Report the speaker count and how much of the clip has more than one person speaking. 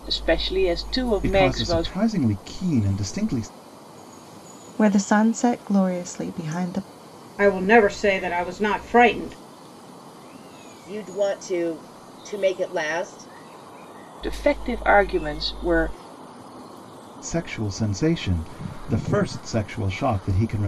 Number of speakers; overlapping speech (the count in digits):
5, about 4%